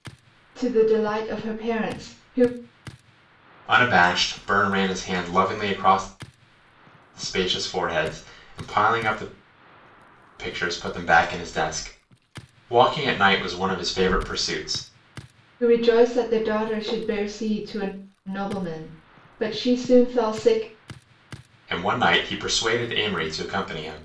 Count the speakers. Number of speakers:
2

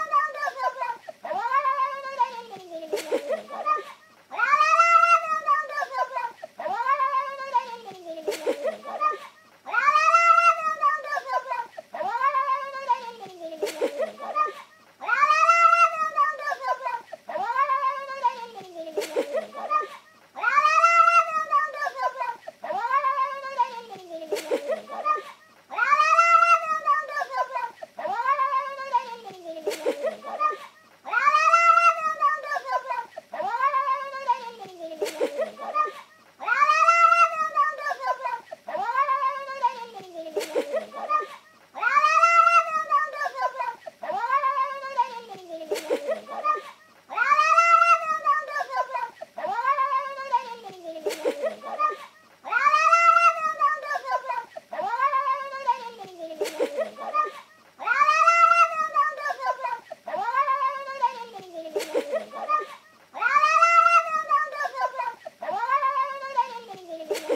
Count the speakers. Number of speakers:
0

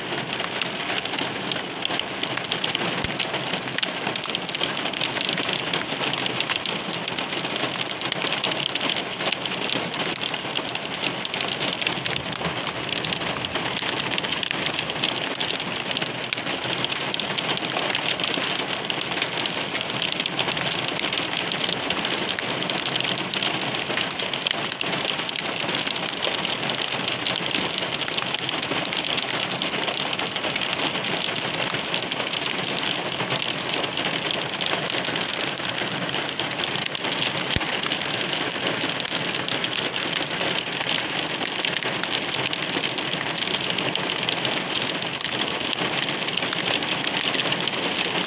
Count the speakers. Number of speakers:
0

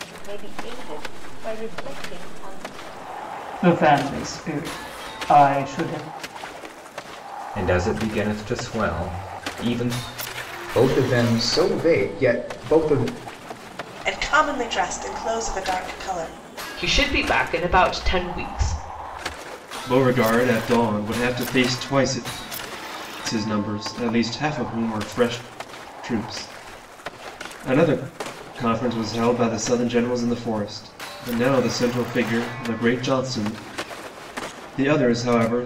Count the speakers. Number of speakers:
7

